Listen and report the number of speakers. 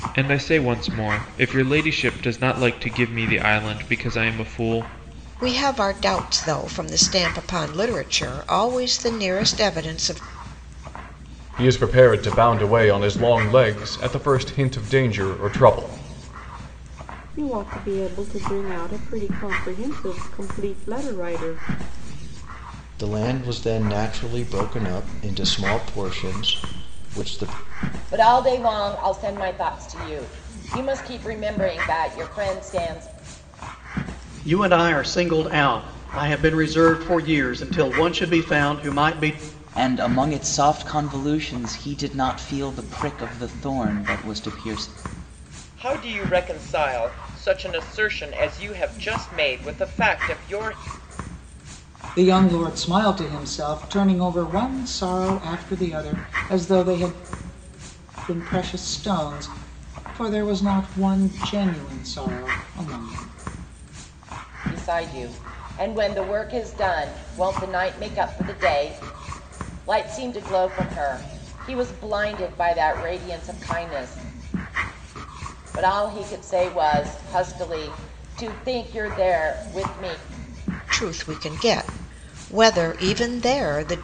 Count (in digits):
10